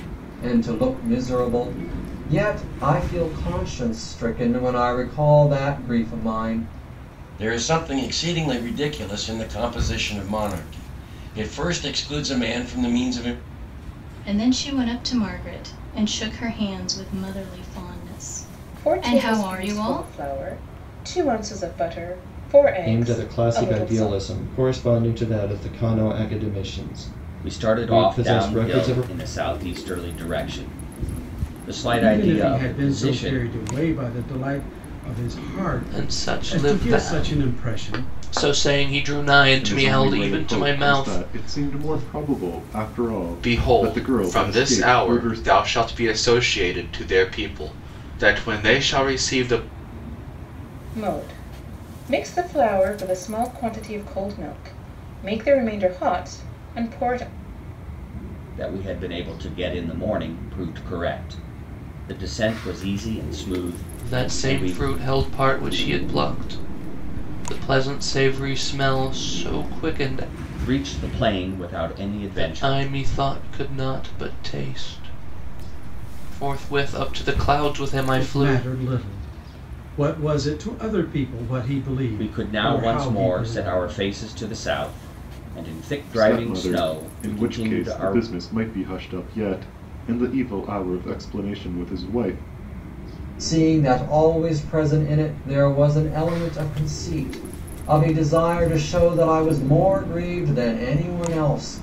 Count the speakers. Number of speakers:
ten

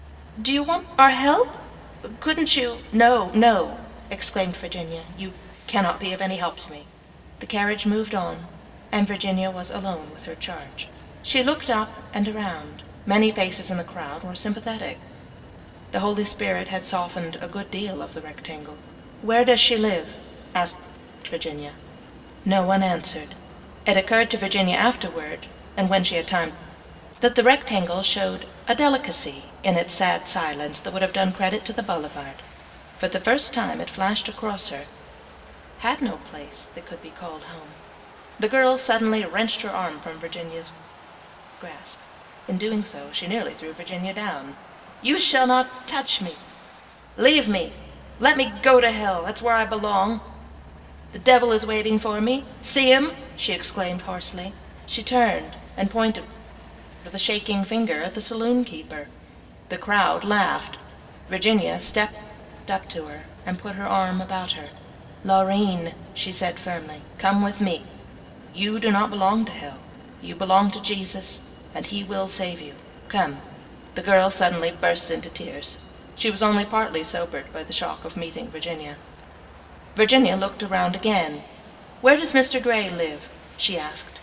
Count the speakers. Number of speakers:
one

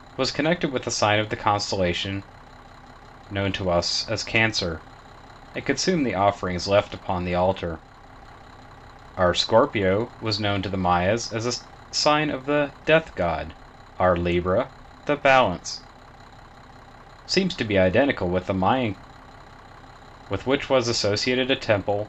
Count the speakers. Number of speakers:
one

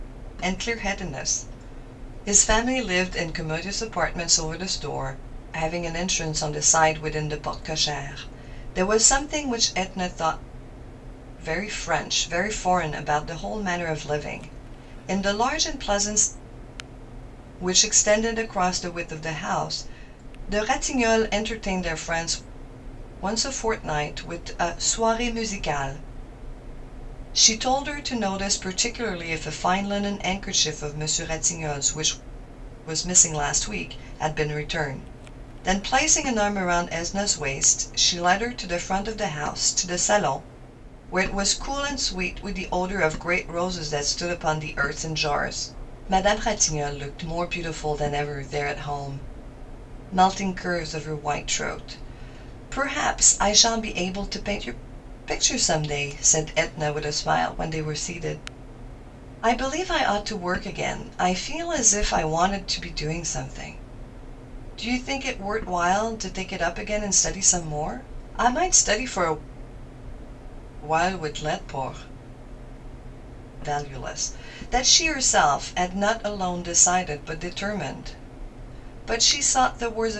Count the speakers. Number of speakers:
one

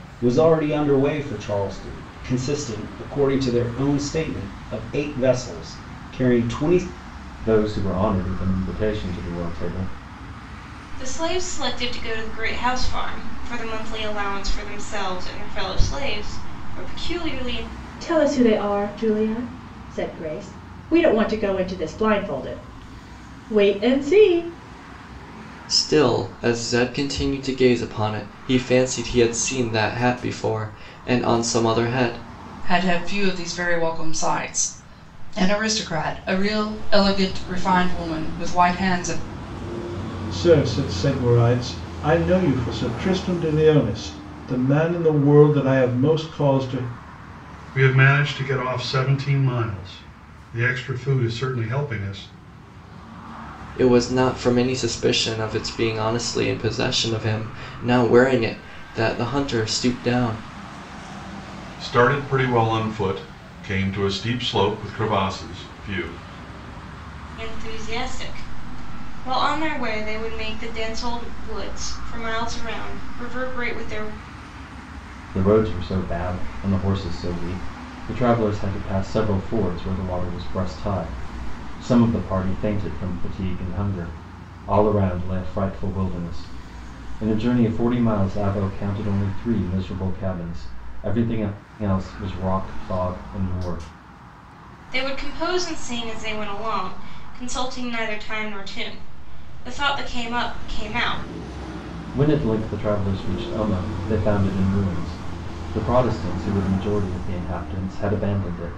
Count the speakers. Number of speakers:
eight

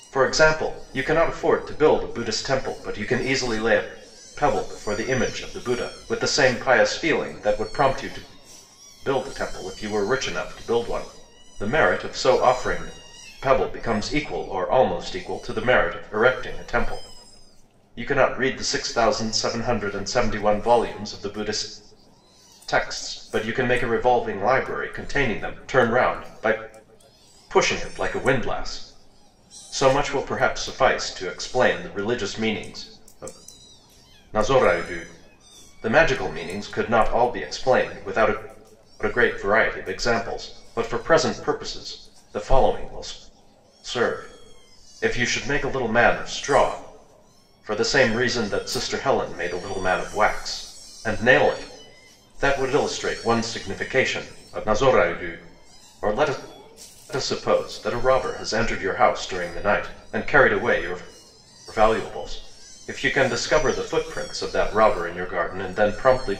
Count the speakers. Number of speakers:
one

